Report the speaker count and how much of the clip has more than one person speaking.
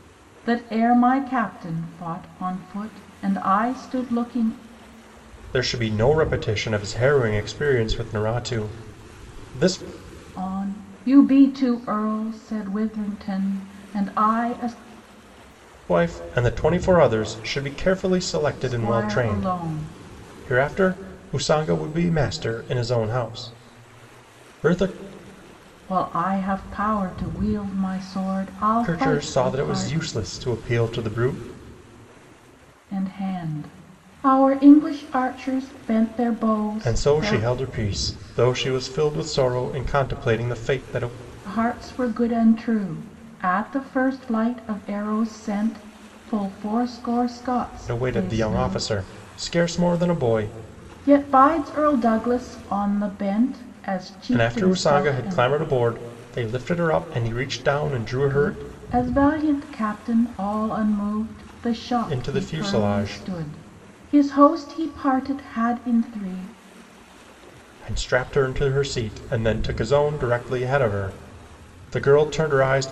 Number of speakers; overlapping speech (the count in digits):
2, about 9%